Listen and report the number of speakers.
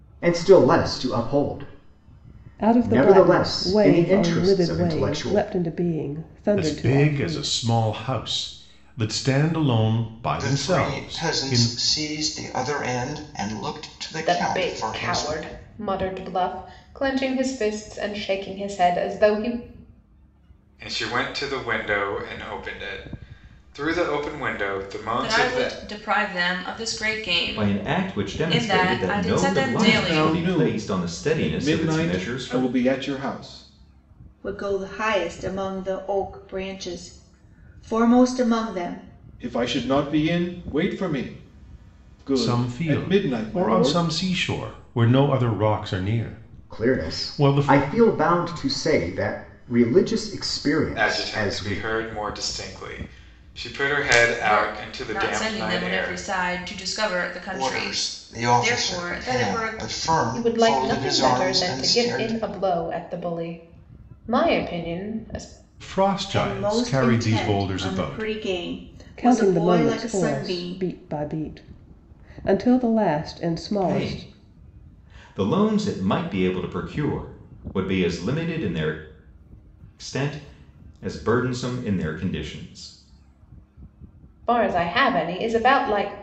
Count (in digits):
10